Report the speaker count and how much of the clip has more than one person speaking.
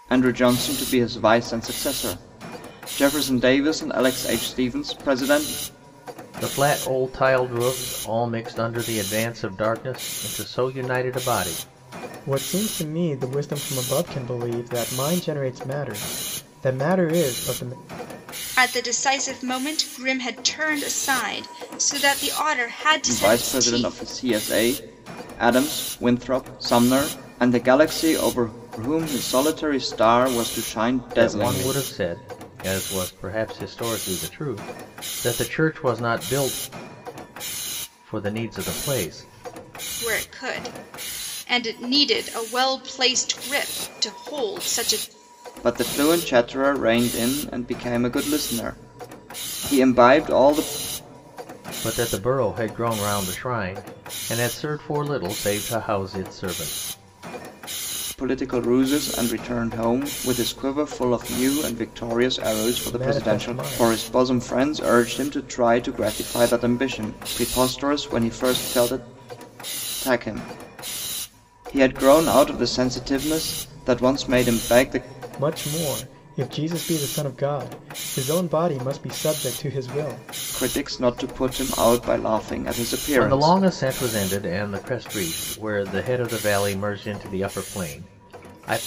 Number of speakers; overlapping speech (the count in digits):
4, about 4%